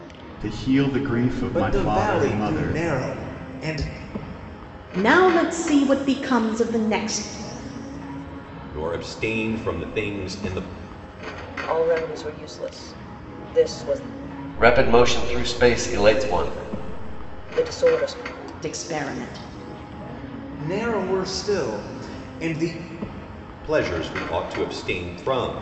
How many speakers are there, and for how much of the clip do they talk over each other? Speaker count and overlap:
6, about 8%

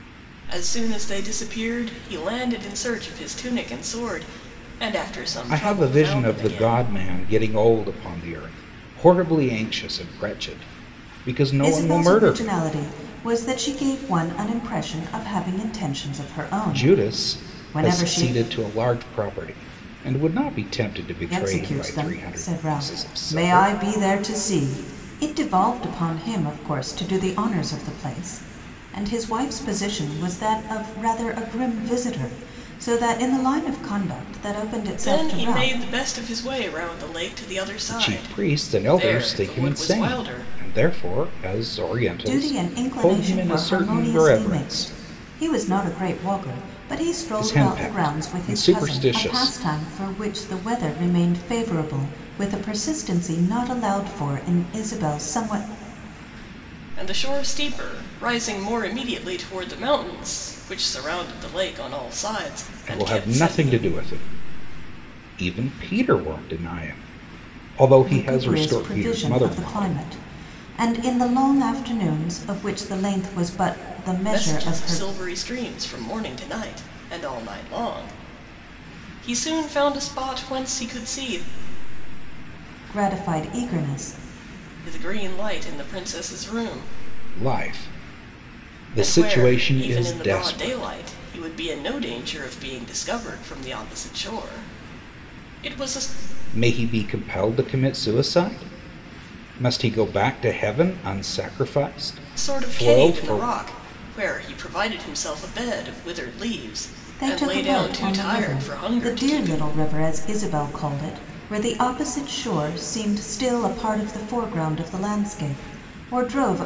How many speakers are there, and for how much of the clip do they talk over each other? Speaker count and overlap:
3, about 21%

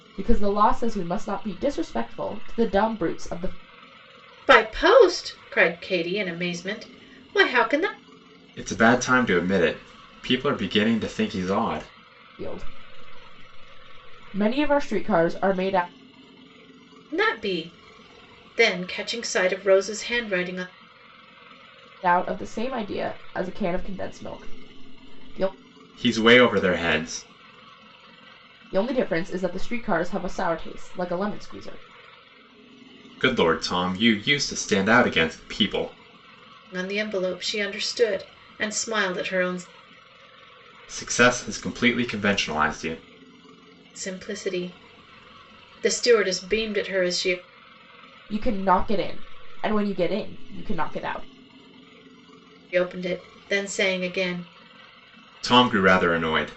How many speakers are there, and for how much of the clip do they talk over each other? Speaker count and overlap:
3, no overlap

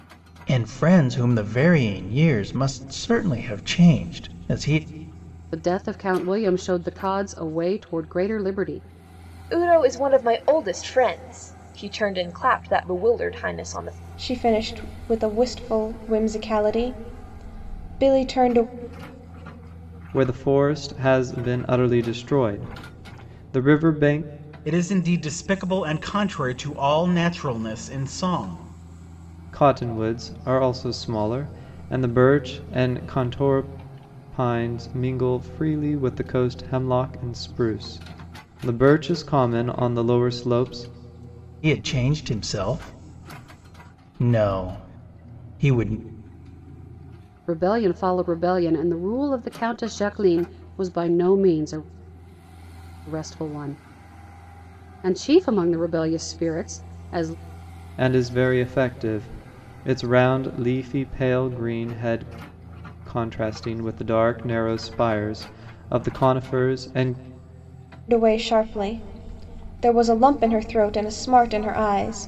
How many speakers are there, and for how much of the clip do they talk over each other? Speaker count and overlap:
6, no overlap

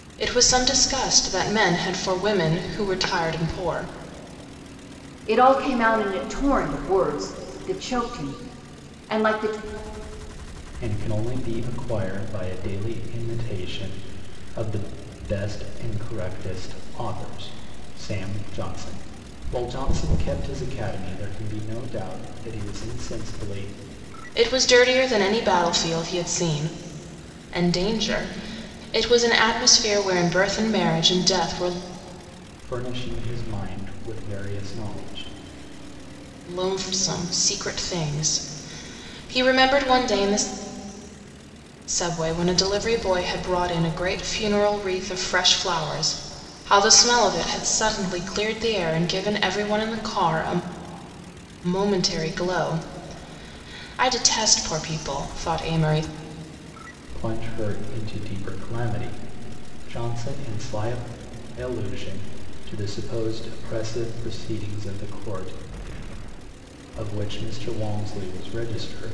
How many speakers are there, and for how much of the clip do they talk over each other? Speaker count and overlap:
3, no overlap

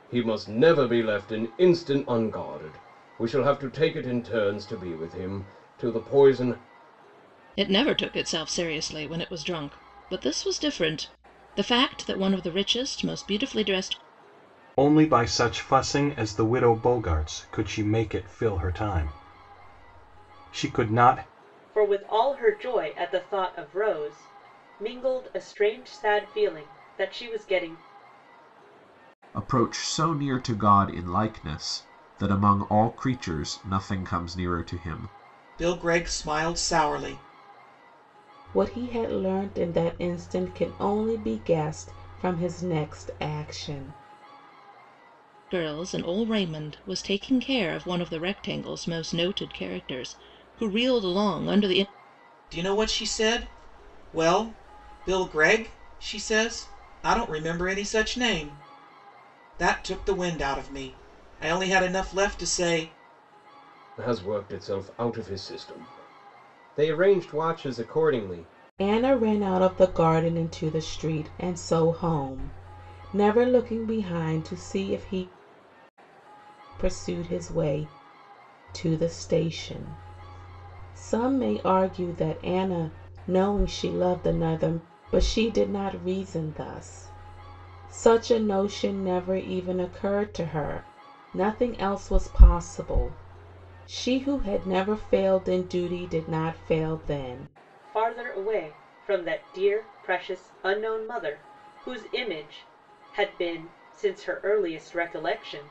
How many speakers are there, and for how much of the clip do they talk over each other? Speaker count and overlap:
7, no overlap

